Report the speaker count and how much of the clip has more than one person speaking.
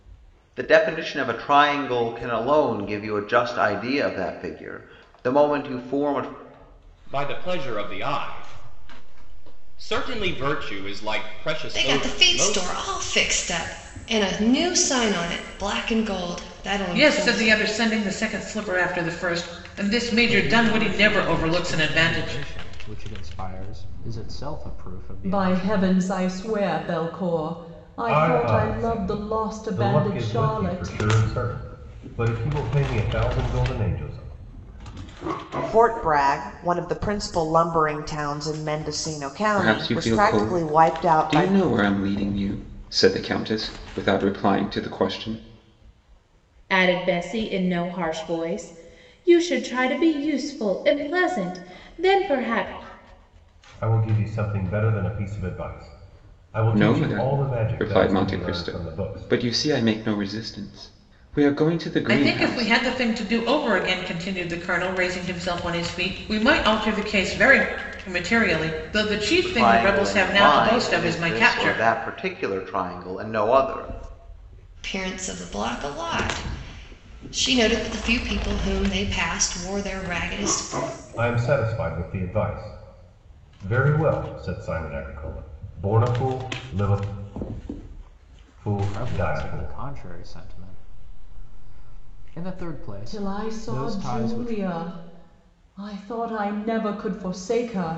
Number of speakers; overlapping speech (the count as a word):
ten, about 18%